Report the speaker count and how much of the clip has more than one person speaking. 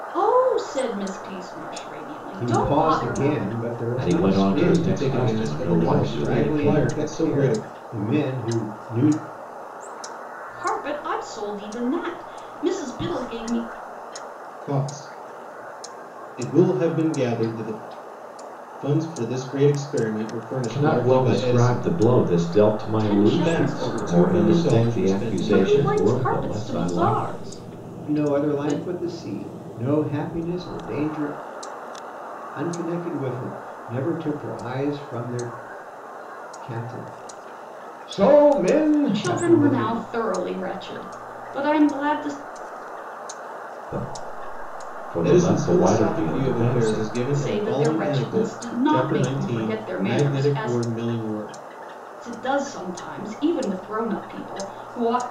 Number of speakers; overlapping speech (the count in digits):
4, about 32%